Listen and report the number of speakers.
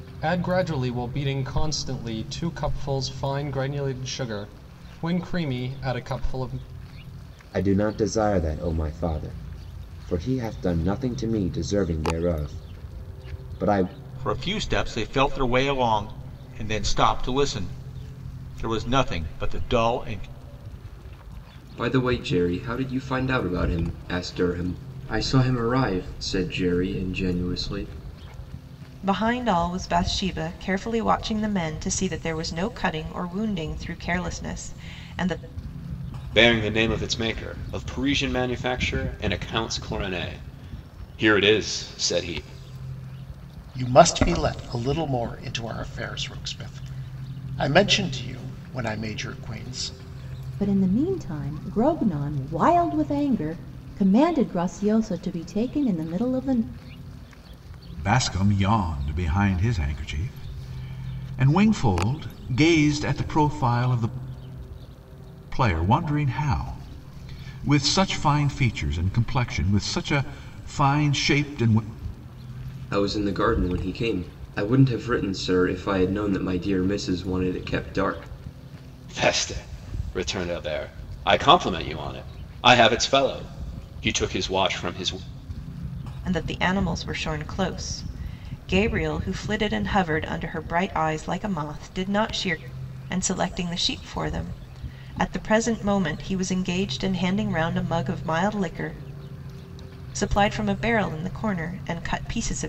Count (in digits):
9